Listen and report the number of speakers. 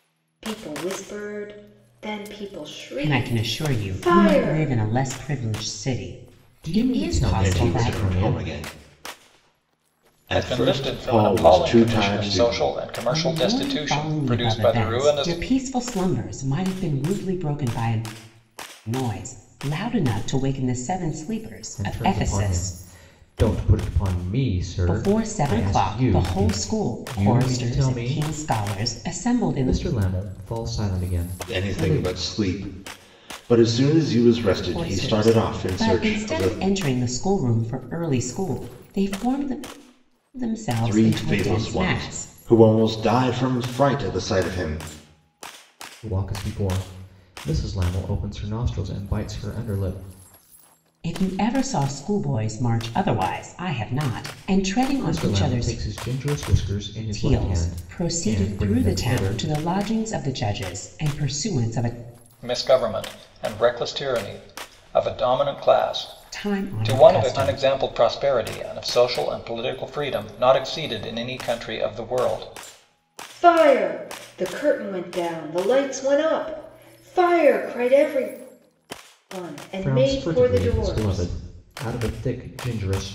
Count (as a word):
five